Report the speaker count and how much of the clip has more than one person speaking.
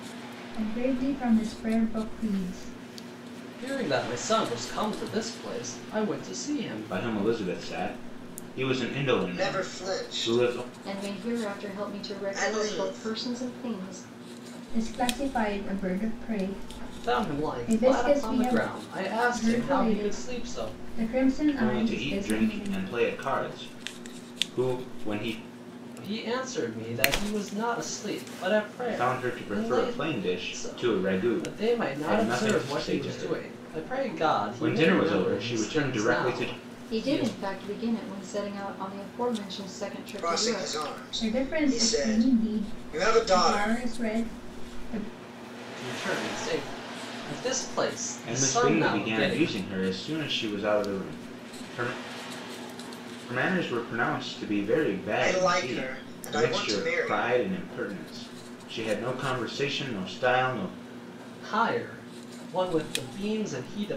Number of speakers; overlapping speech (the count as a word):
five, about 36%